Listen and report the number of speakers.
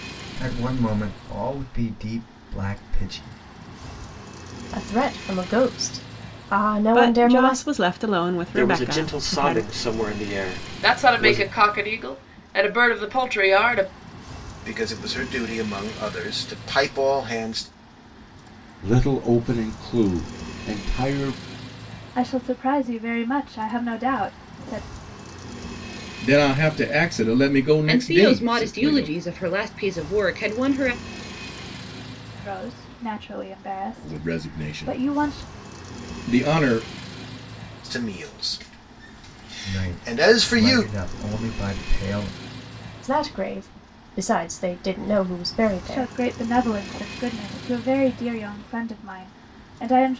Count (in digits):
10